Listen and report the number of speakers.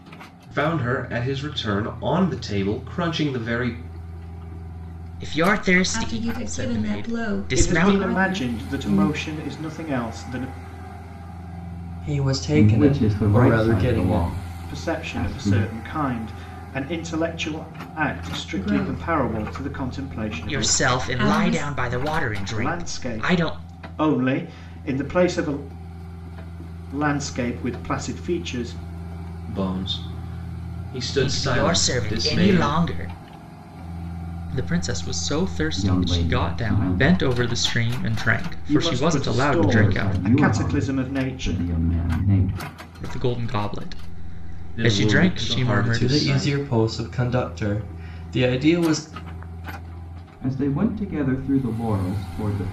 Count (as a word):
six